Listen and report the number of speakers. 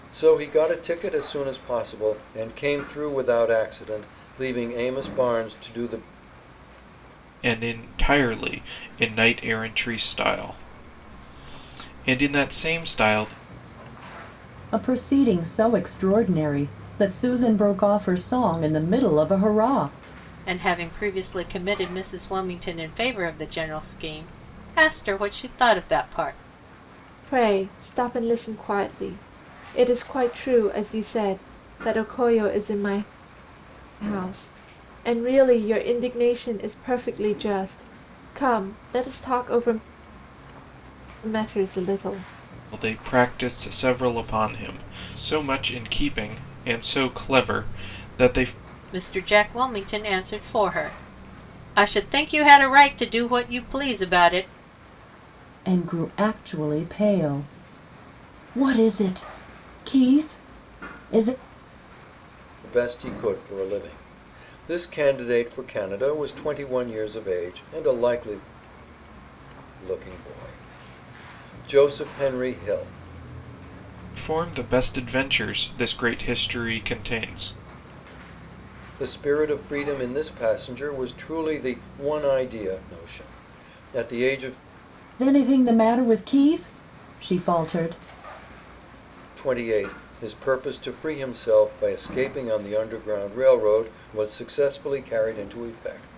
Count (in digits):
5